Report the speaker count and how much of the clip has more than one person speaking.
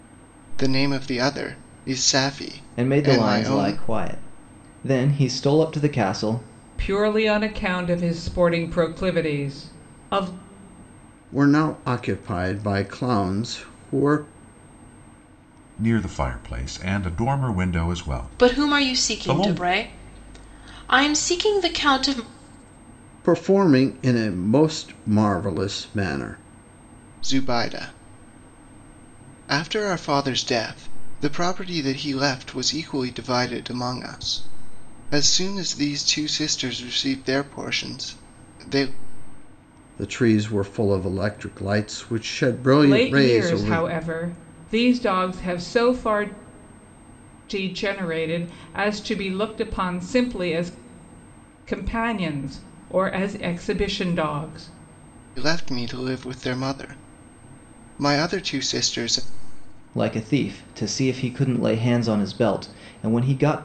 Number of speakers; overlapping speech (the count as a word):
six, about 5%